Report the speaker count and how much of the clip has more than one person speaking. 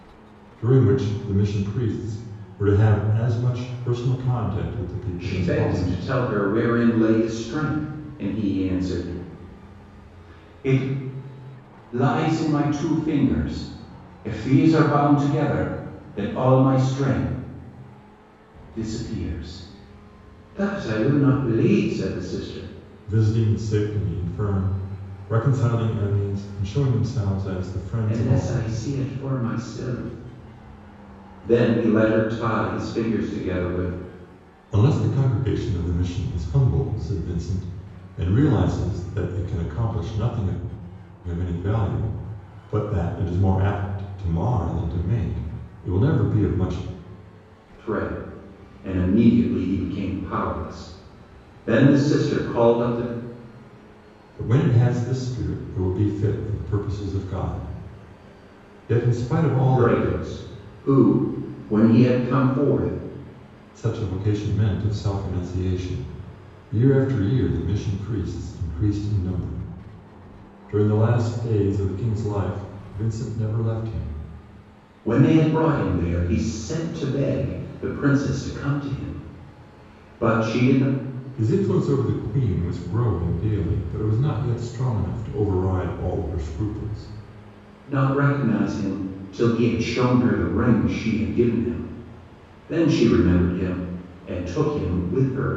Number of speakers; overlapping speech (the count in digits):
2, about 2%